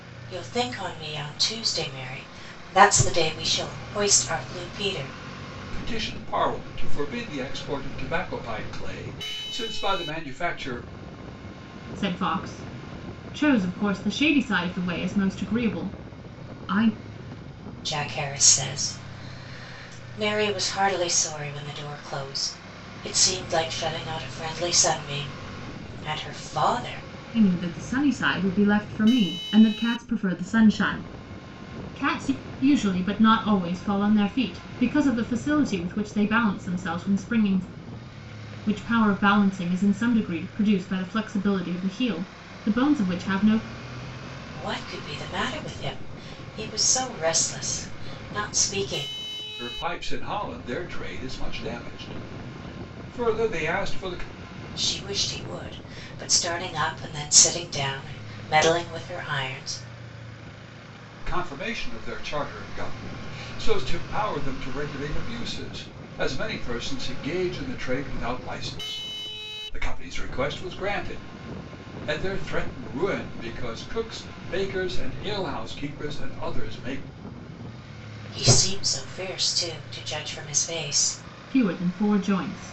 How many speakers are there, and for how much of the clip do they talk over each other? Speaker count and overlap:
3, no overlap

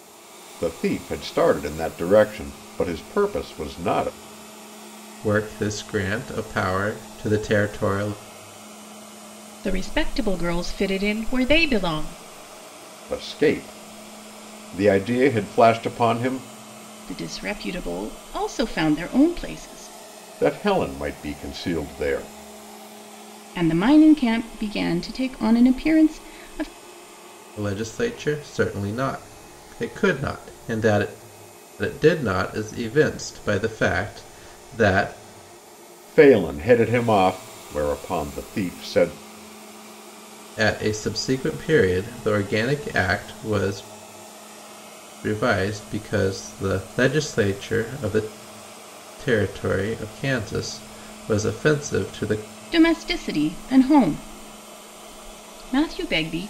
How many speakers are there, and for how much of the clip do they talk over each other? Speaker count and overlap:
3, no overlap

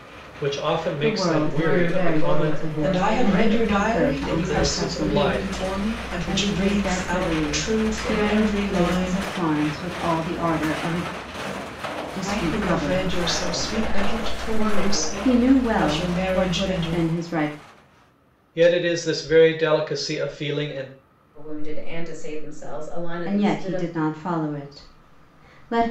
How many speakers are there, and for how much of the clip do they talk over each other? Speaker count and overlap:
4, about 51%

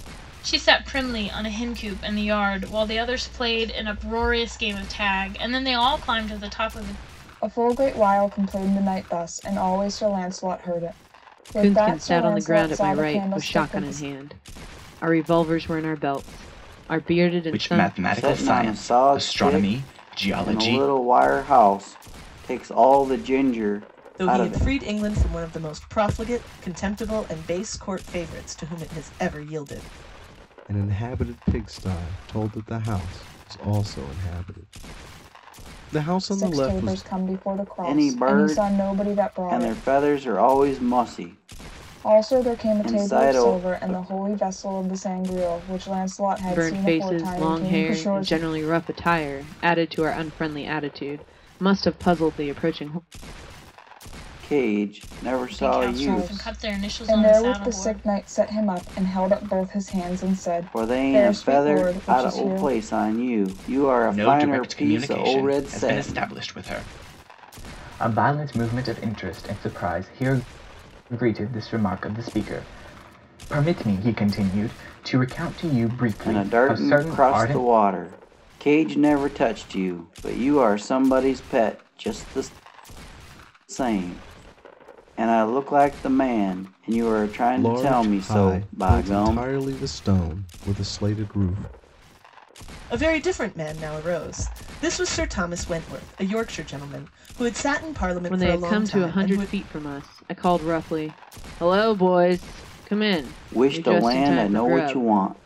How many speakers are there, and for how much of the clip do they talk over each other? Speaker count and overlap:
7, about 25%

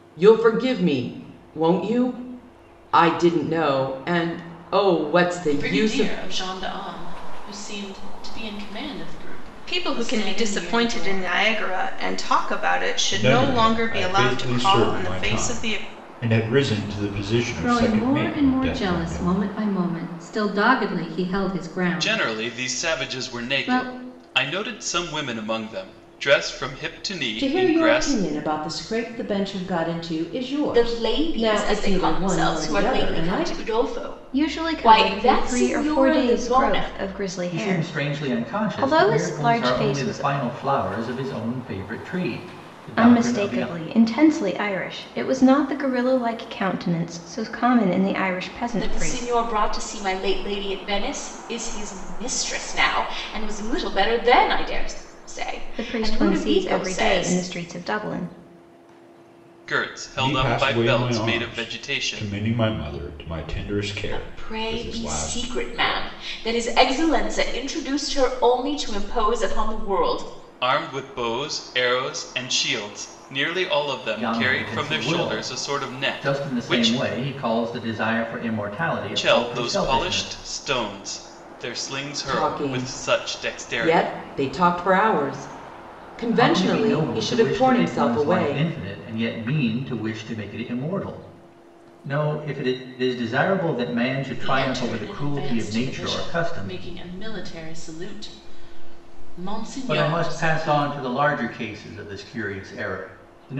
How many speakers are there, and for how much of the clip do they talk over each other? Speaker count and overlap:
10, about 36%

